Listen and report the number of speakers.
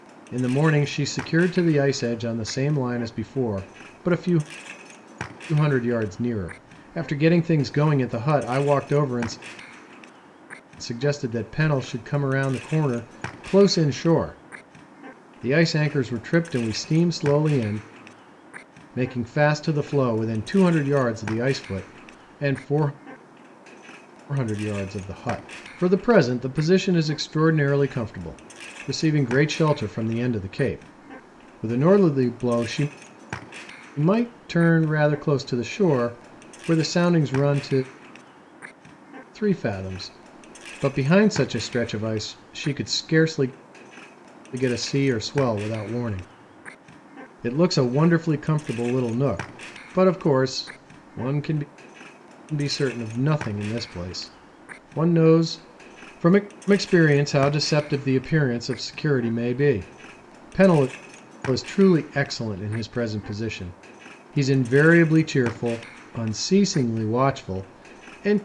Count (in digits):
1